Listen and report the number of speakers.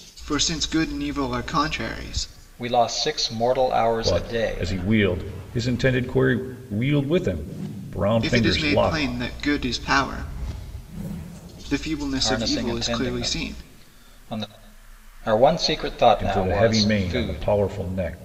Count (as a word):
three